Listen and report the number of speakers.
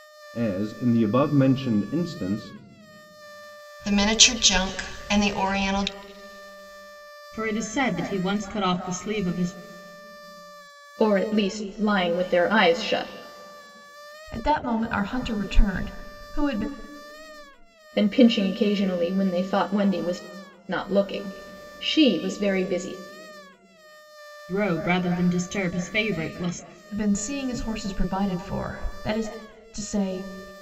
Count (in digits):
5